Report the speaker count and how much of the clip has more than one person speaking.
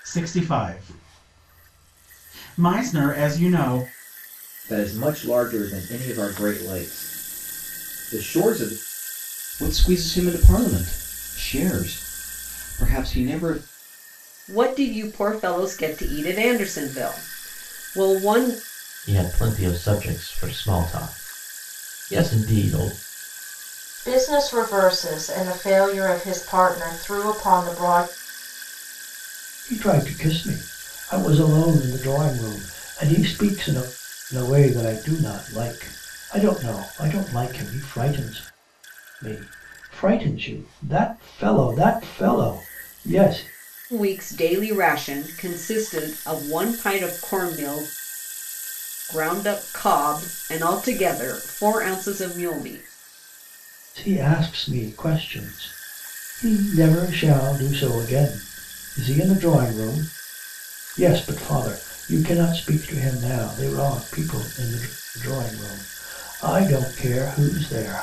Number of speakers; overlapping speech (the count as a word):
seven, no overlap